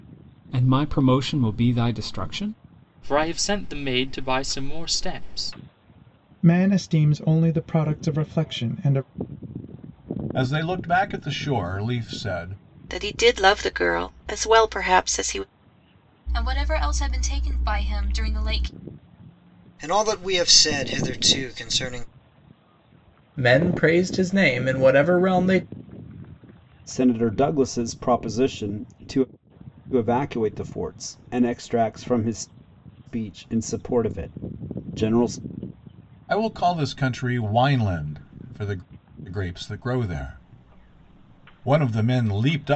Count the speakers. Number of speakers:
9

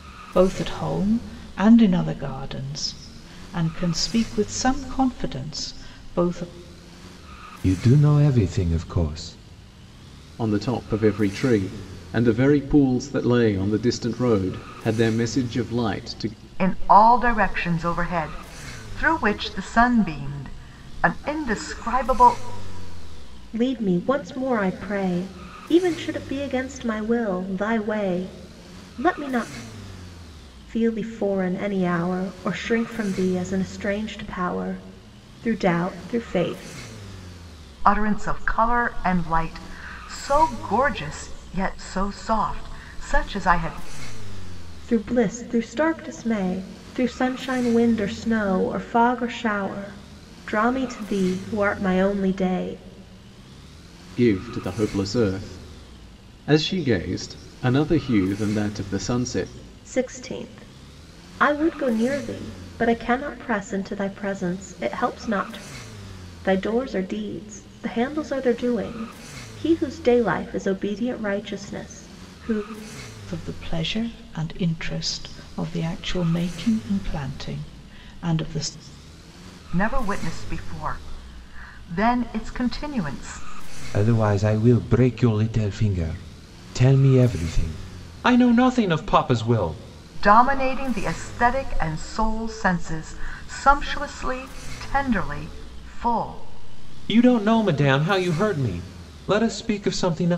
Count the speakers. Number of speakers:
5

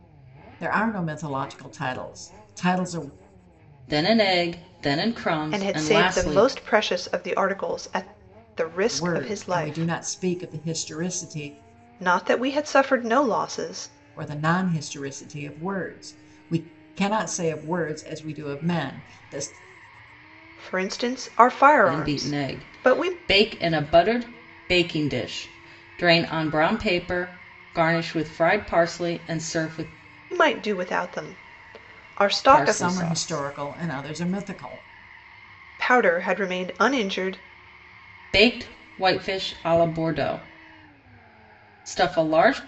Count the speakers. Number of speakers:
3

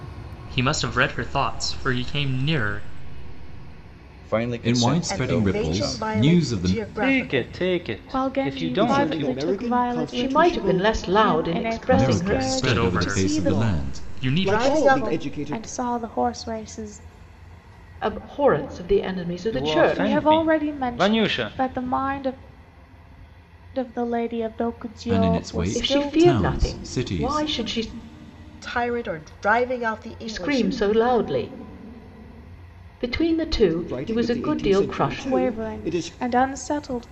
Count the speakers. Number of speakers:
8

